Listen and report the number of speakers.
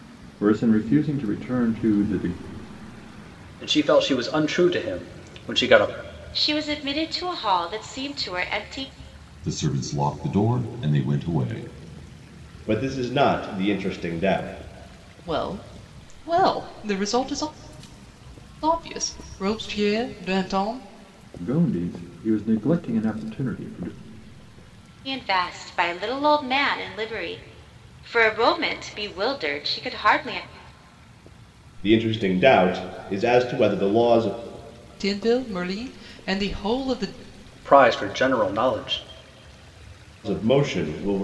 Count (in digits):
6